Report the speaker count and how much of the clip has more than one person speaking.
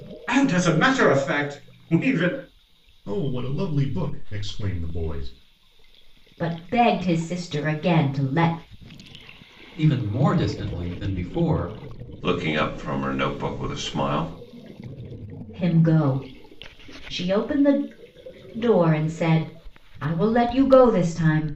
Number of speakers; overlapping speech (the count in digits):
5, no overlap